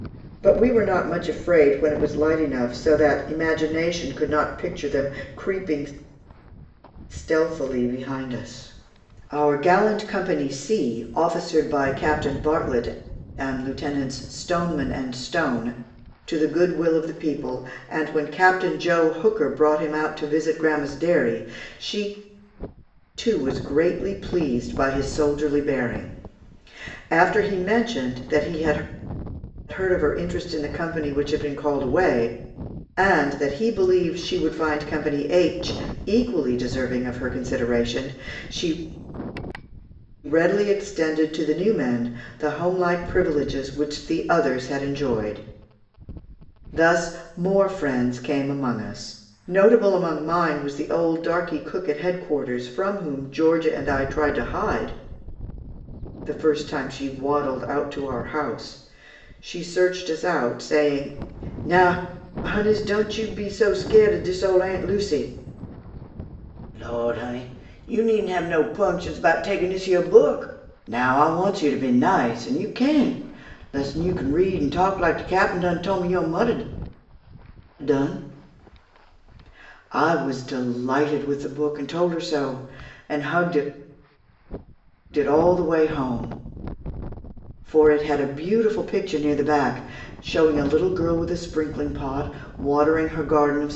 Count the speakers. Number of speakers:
1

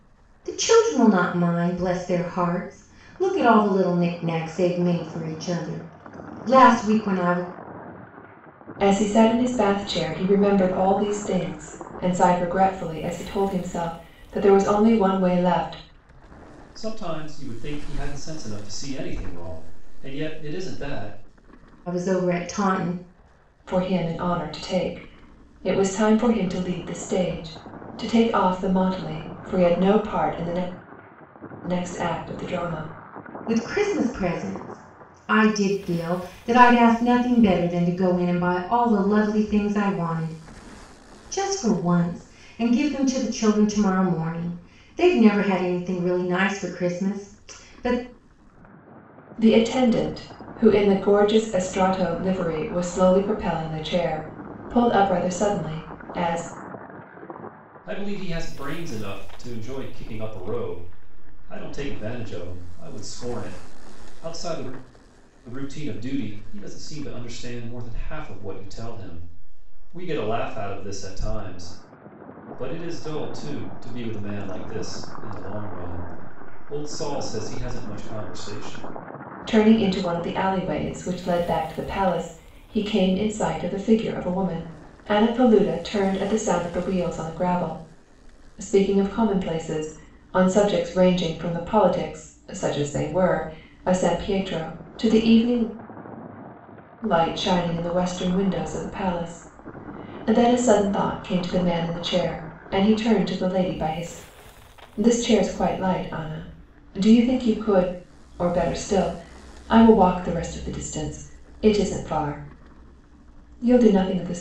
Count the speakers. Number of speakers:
3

